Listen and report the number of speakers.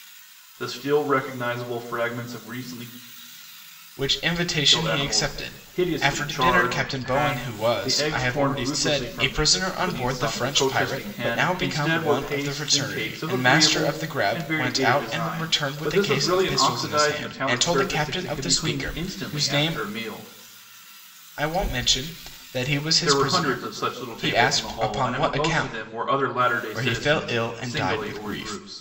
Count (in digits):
2